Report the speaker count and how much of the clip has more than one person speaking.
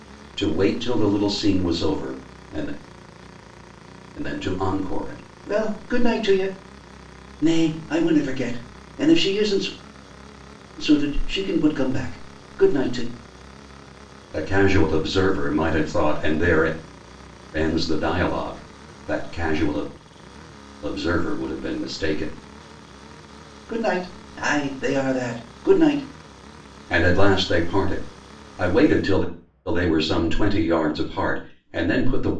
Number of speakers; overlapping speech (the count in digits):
1, no overlap